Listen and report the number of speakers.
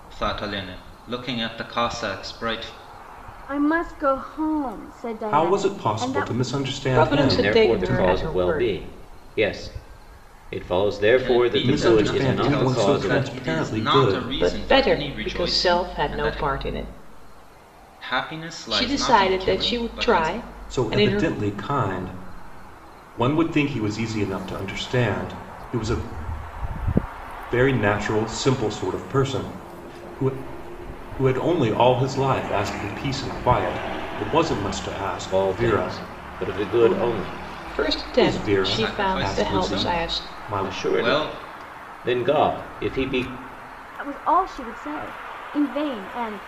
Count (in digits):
5